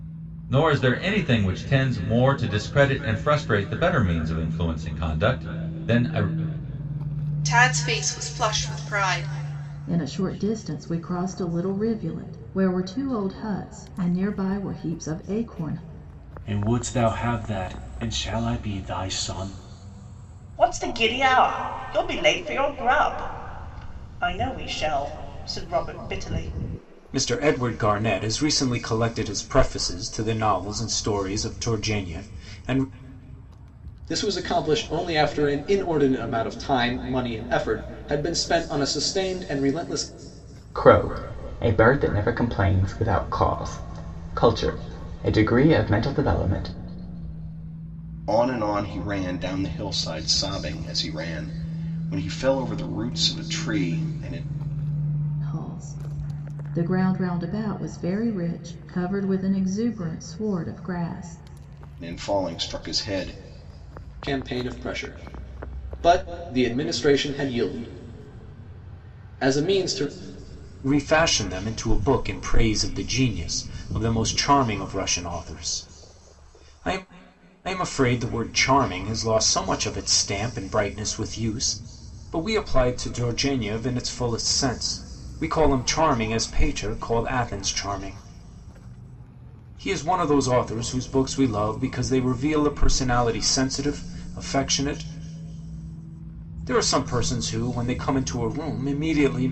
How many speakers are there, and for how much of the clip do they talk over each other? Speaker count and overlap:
nine, no overlap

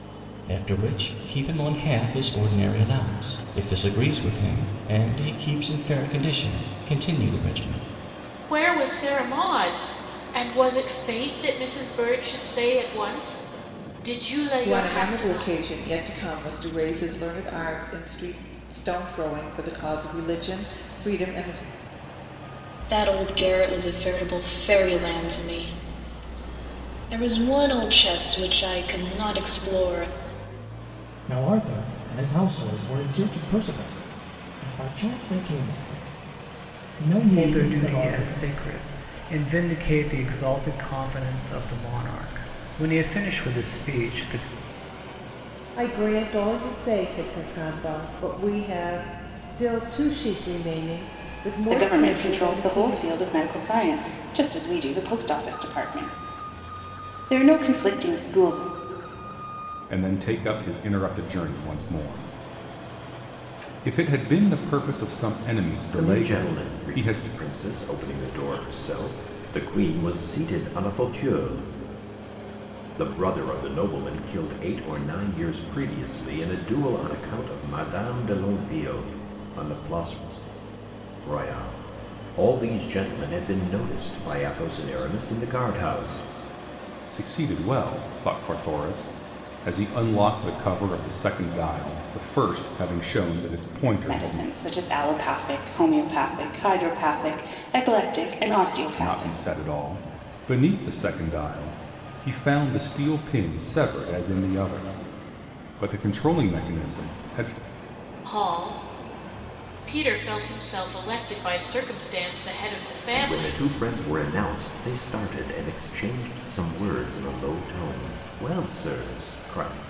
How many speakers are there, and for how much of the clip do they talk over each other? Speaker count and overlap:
ten, about 5%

